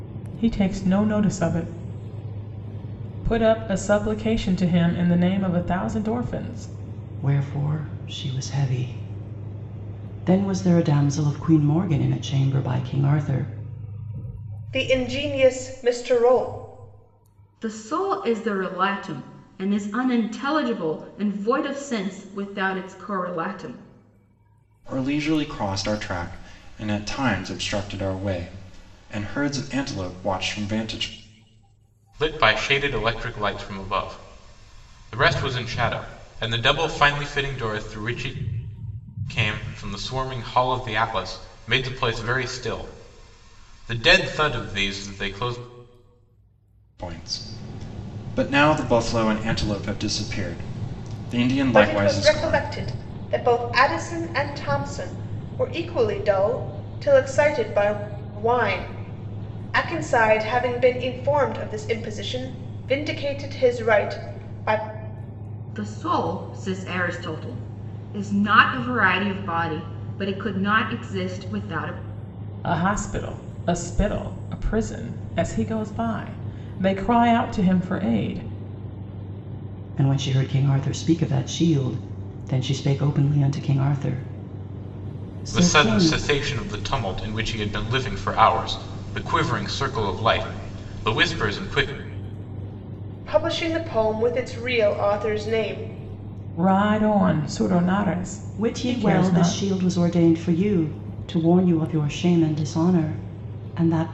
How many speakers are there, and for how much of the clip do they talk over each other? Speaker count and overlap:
6, about 3%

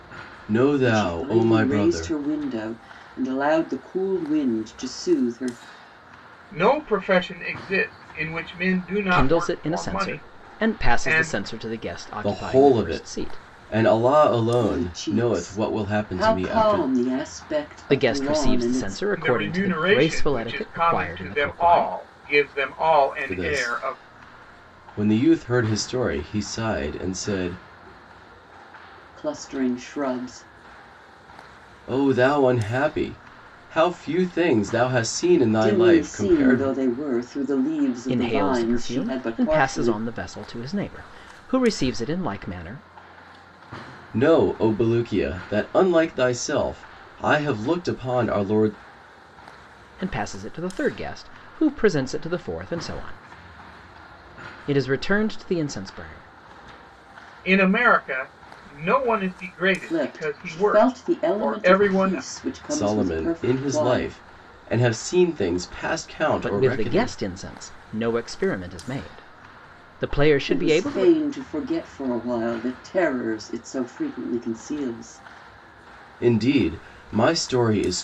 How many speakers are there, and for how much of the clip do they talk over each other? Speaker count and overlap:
4, about 26%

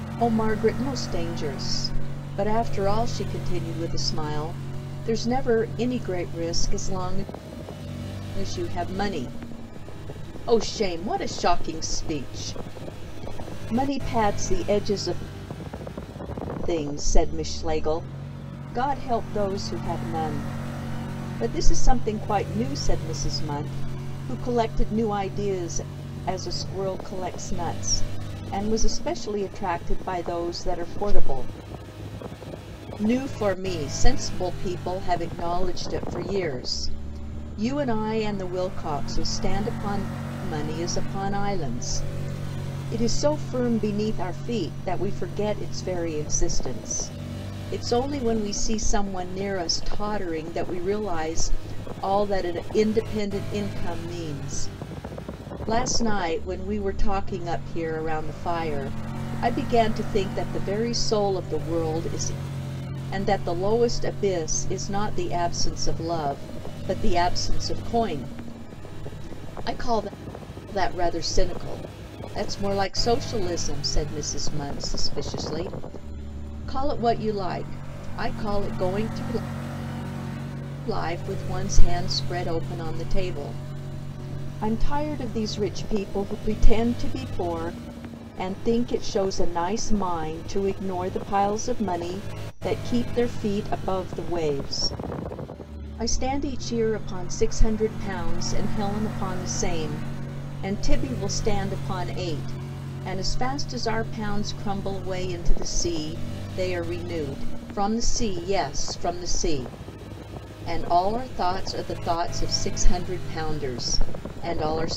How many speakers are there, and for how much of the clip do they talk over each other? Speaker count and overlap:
1, no overlap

